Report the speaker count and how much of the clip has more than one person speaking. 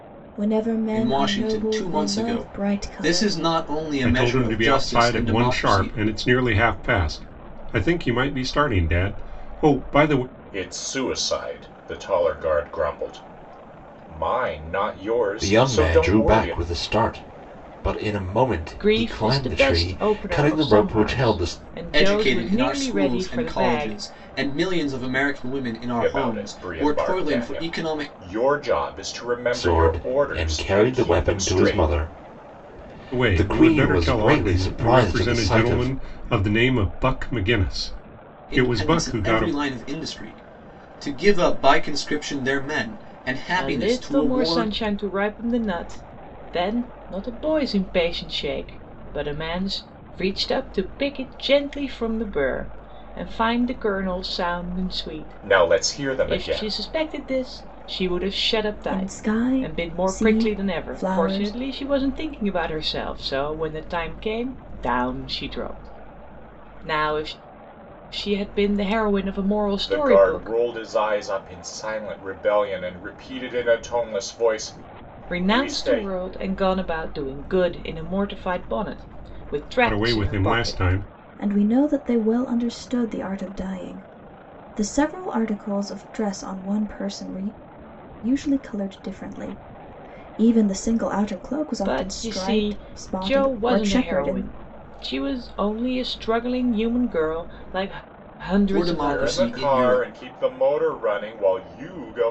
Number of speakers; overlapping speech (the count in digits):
6, about 30%